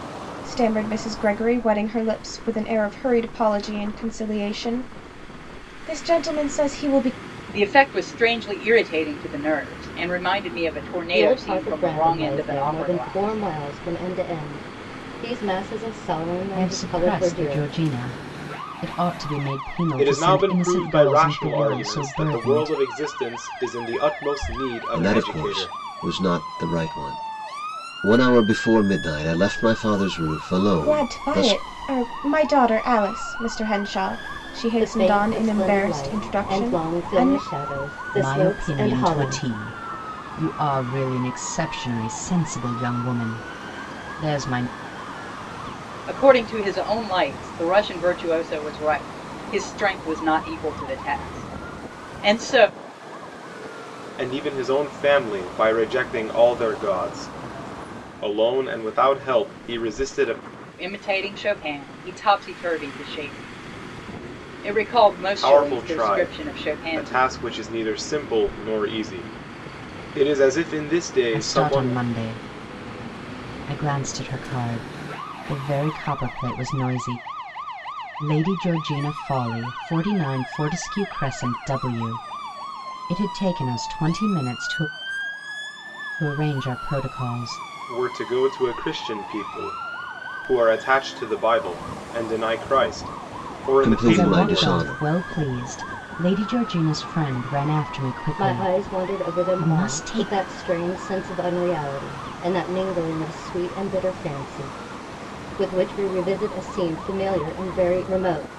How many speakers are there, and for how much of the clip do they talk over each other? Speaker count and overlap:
six, about 17%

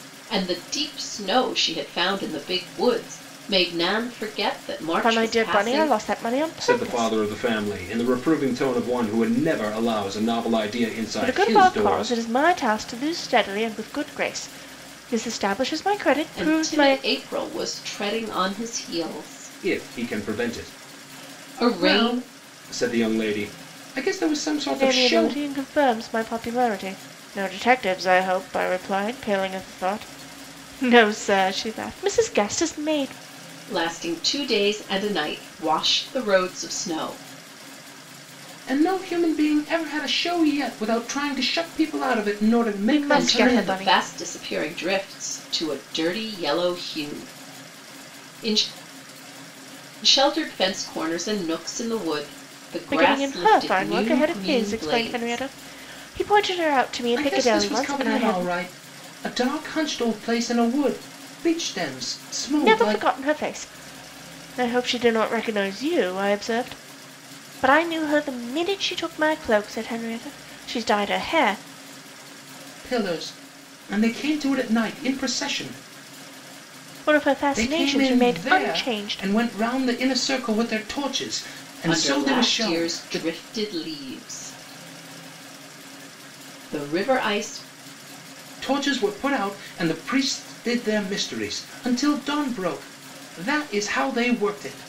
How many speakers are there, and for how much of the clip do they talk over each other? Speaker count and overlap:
three, about 16%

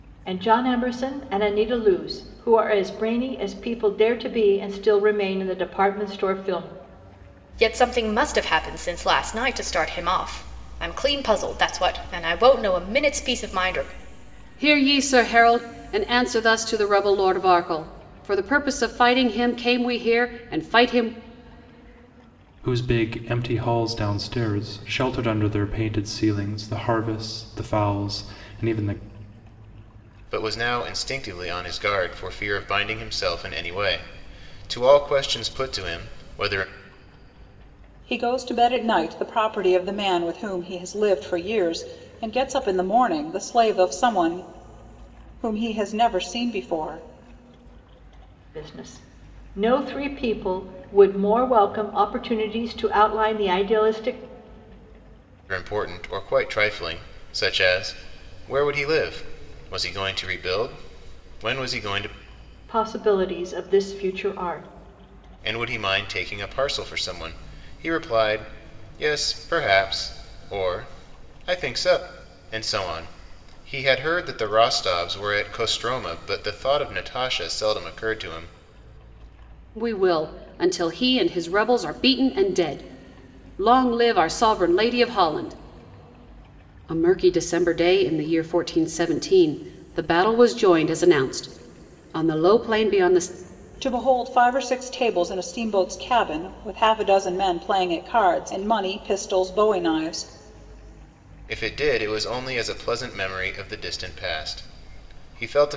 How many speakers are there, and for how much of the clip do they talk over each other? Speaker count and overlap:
six, no overlap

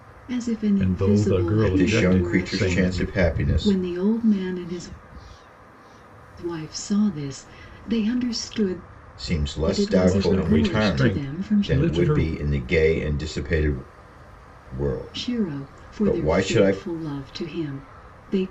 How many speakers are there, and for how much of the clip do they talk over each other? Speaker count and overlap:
three, about 40%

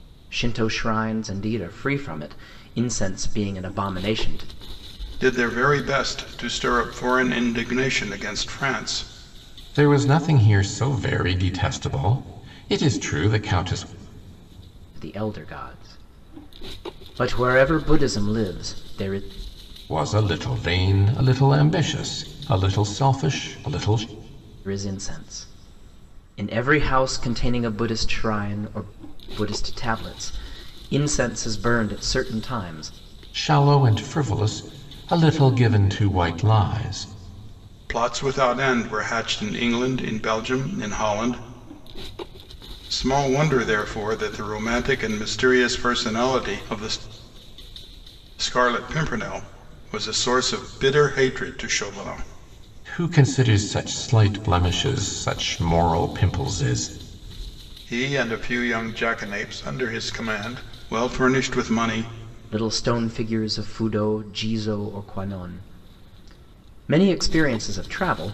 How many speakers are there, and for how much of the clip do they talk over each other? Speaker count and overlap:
three, no overlap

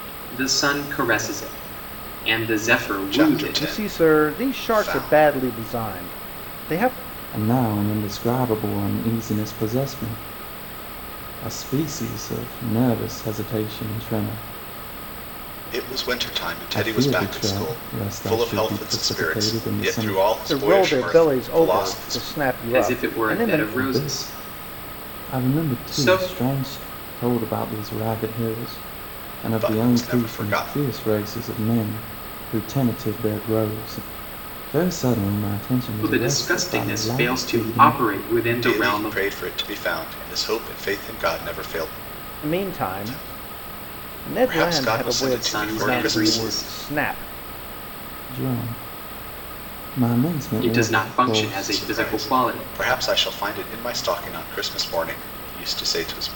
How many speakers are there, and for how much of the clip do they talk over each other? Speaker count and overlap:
four, about 37%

